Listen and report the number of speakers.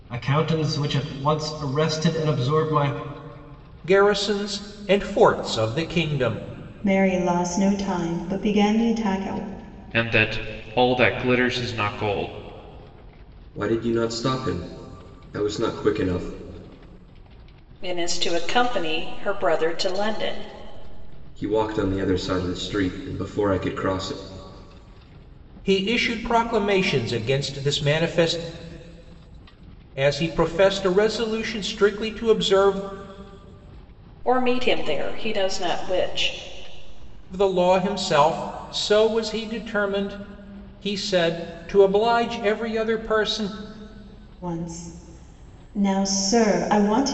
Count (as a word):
six